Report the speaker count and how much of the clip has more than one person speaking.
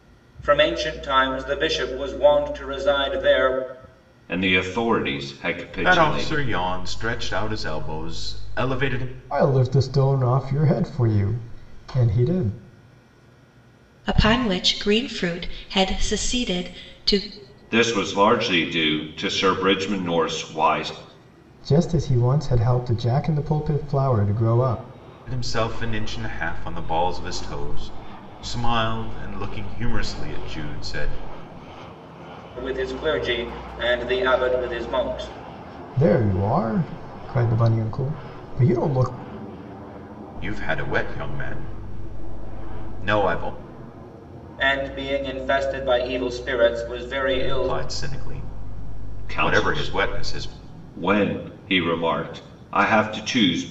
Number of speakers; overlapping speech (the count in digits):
5, about 5%